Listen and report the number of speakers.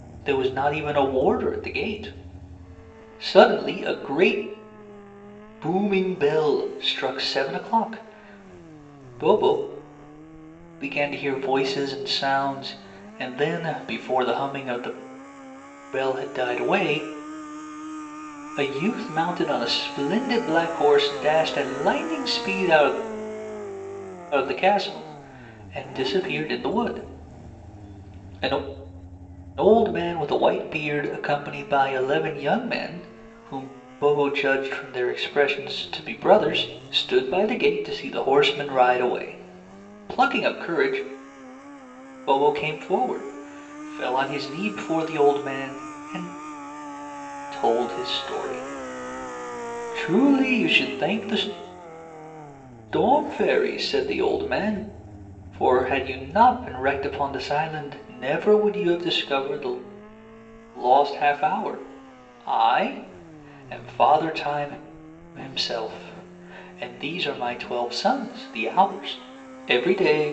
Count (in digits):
1